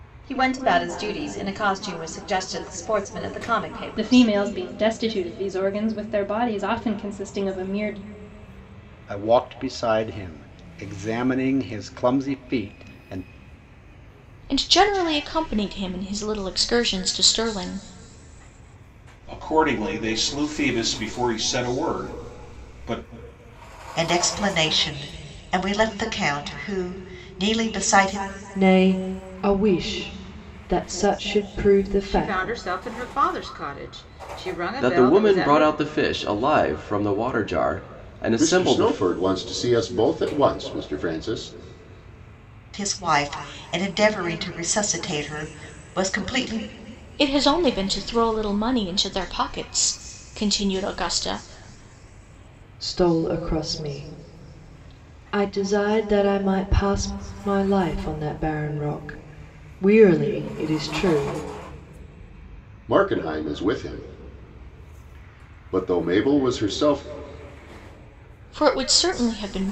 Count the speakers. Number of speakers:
10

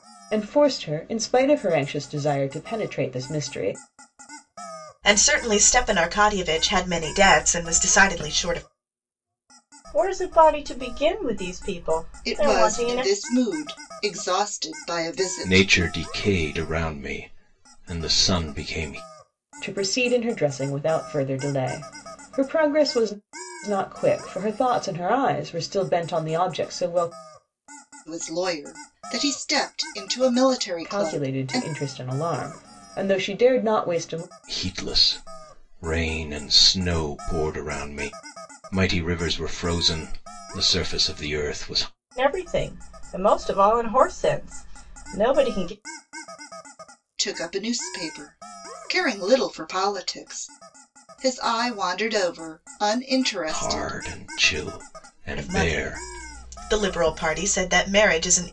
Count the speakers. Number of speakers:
5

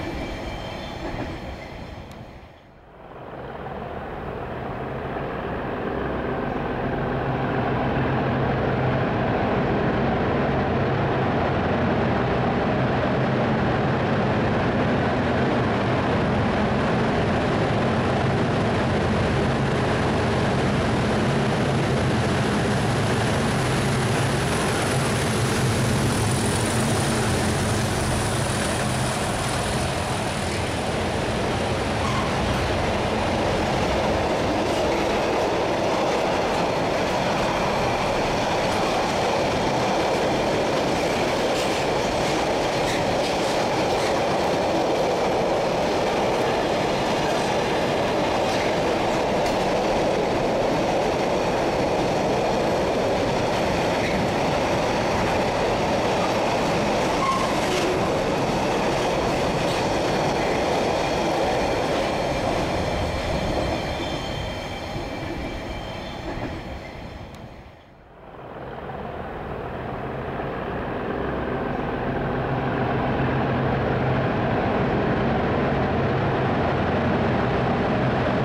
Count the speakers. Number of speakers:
0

